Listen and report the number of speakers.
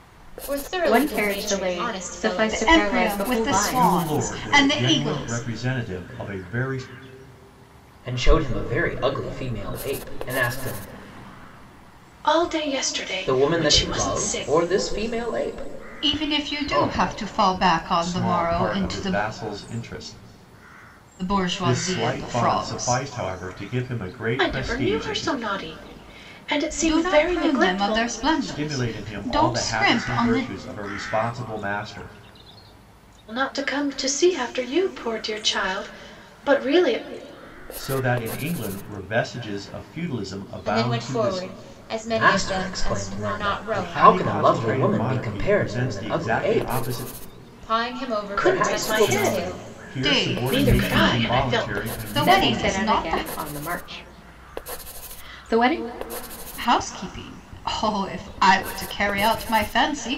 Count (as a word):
six